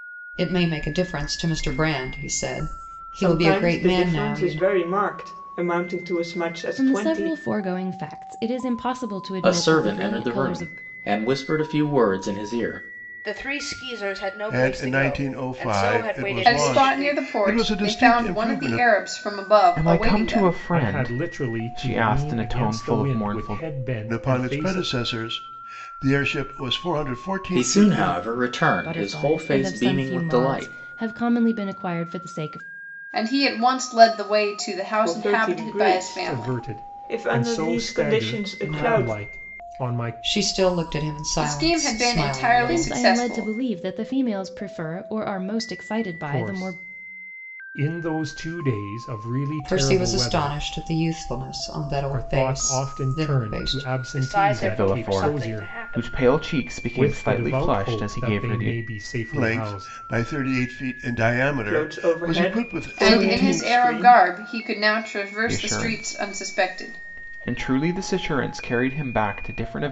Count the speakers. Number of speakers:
nine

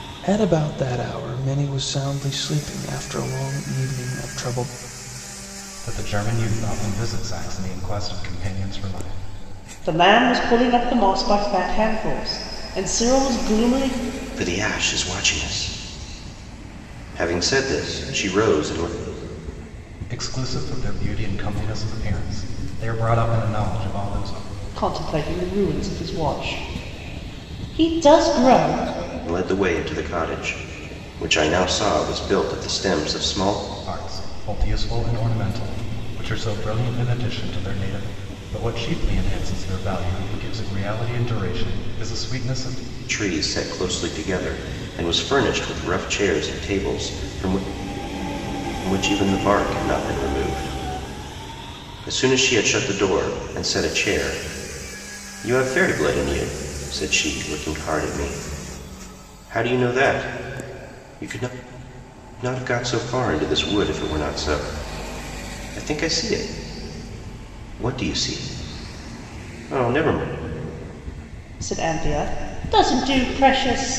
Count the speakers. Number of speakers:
four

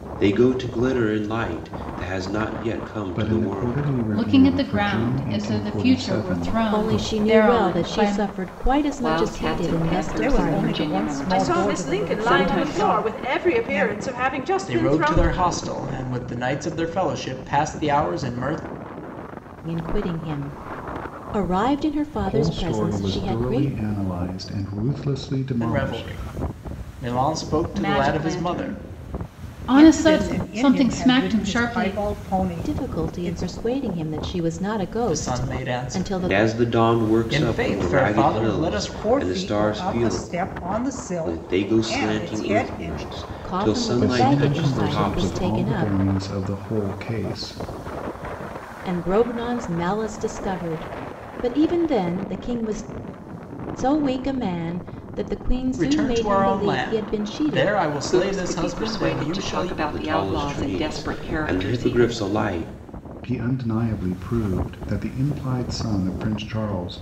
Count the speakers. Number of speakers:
eight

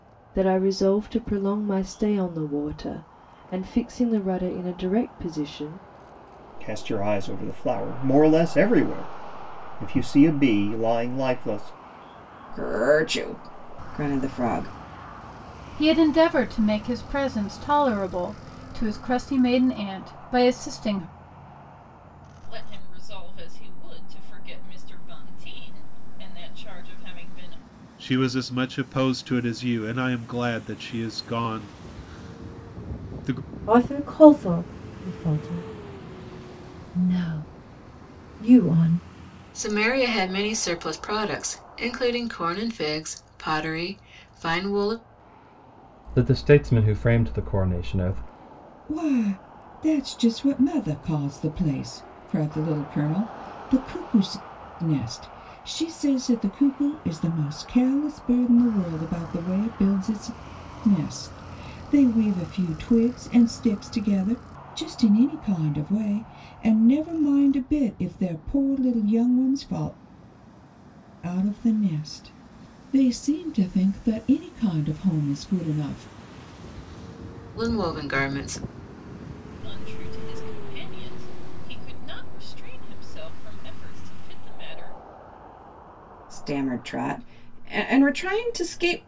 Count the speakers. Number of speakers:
ten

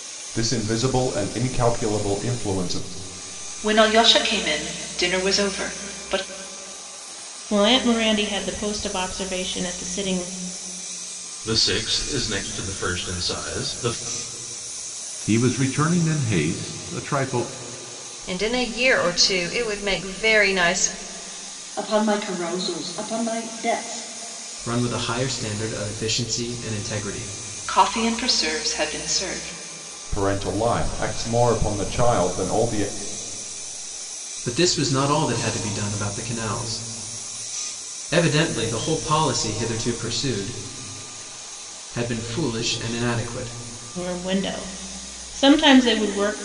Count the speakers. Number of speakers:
eight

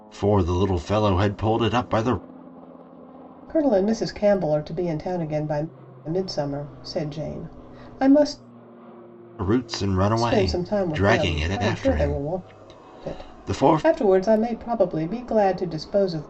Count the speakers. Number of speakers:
two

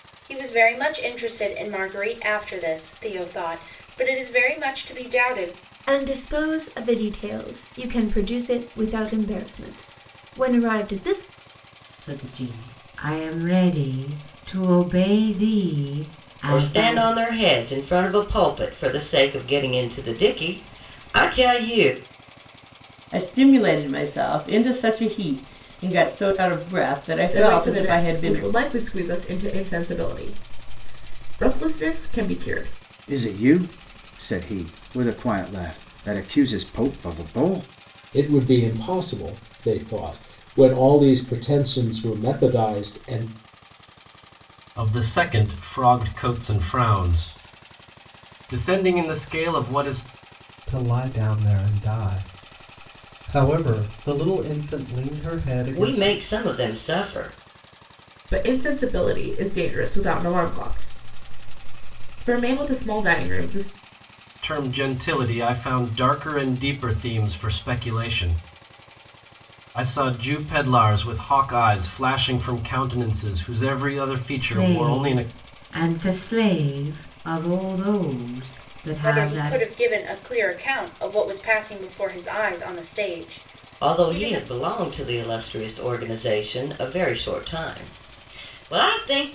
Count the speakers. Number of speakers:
ten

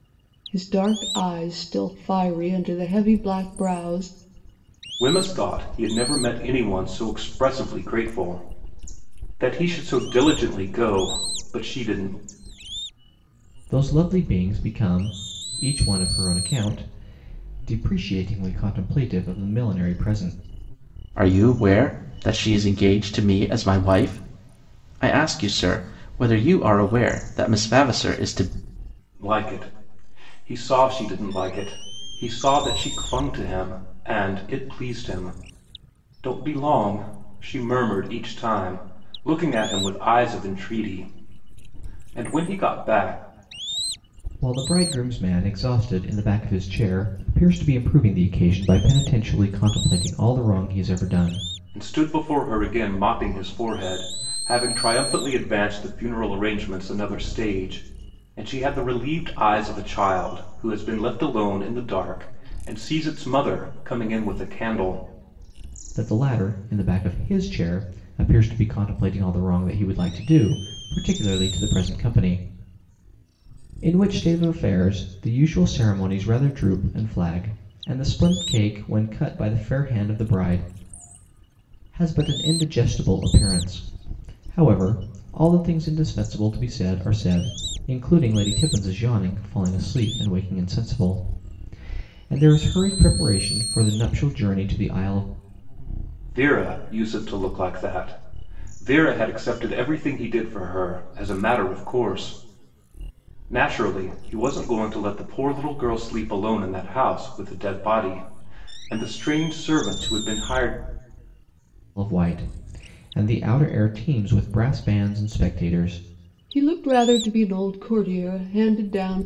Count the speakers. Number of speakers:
four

